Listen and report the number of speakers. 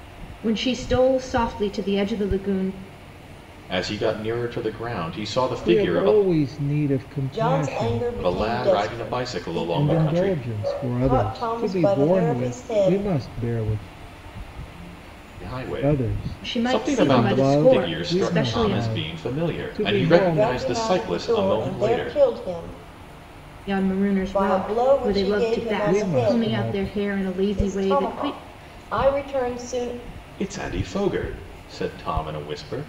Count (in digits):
4